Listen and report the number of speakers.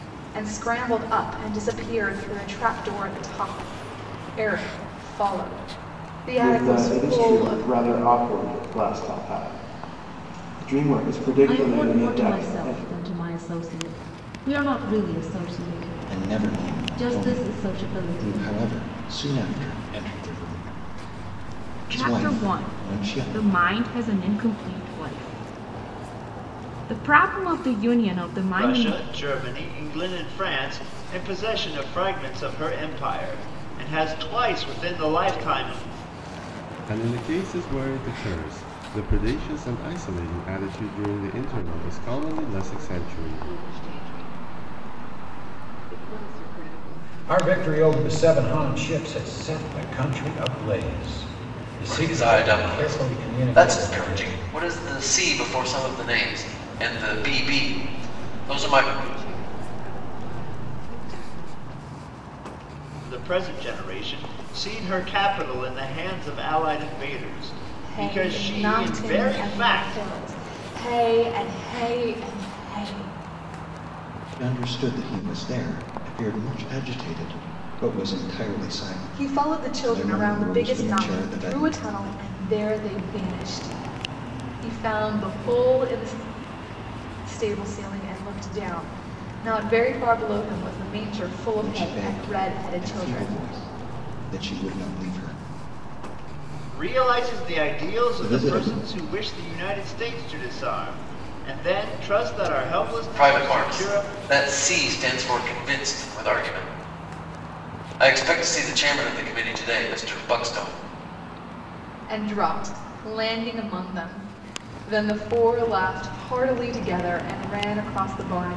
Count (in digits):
10